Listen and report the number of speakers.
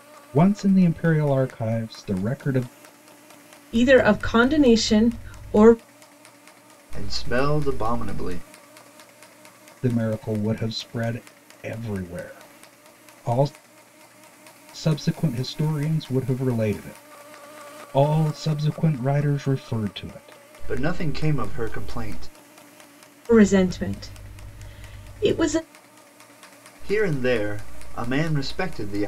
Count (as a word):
three